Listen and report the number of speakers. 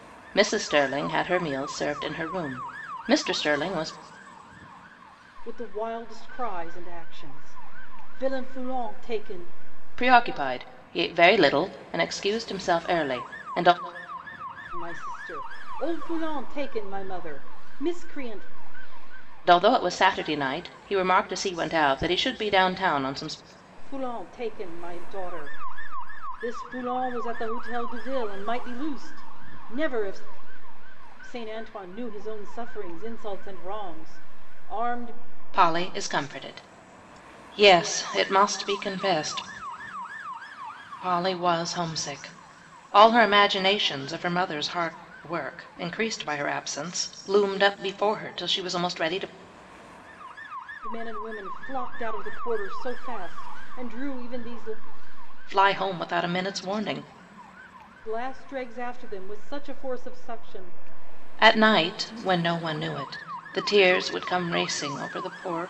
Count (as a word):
two